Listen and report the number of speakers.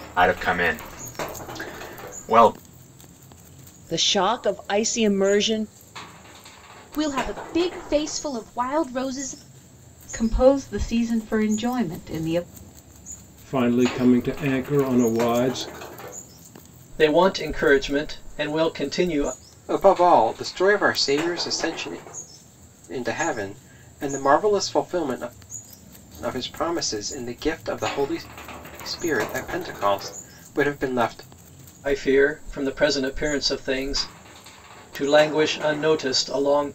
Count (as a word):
seven